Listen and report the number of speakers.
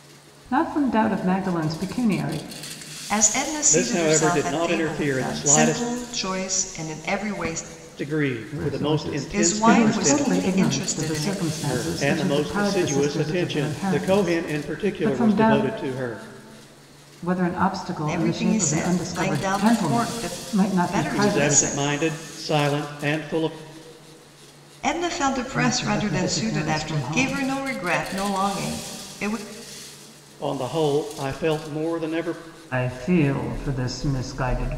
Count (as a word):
three